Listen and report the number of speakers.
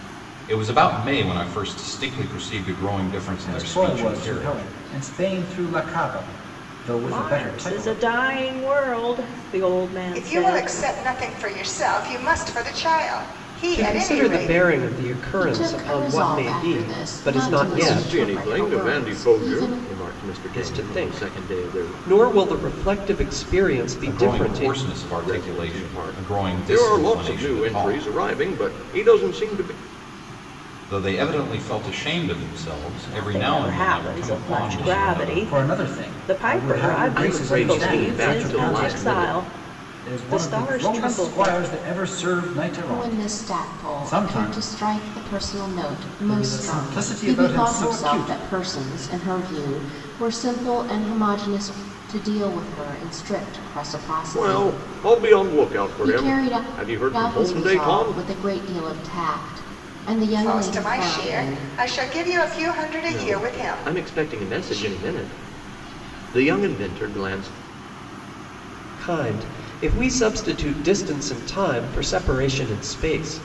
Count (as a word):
seven